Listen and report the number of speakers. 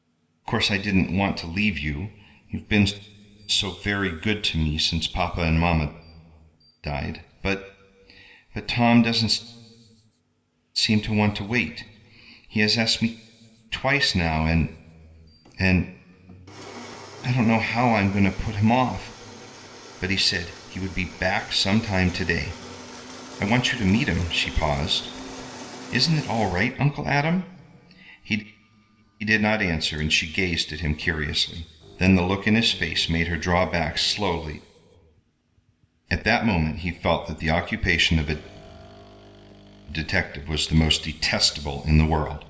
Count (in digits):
1